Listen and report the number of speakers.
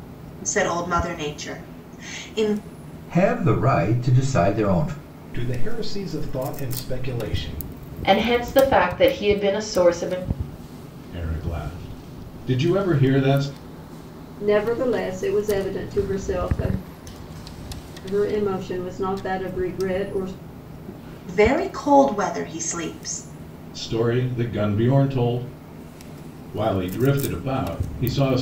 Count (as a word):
six